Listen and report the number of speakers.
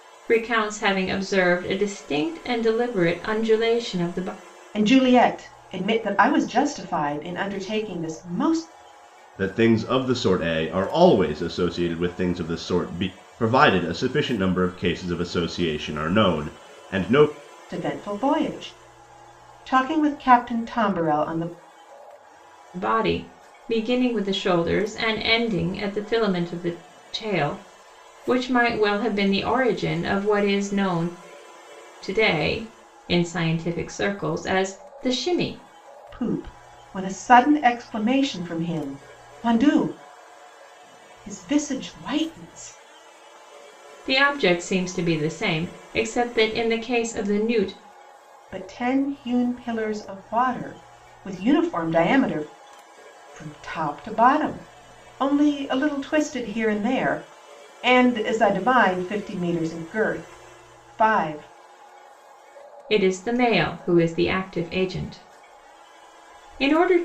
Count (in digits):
3